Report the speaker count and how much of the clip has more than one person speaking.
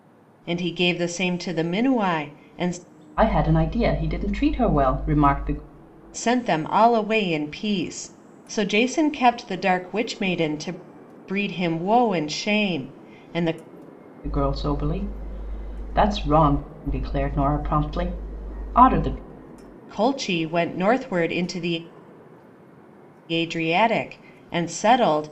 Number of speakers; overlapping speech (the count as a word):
two, no overlap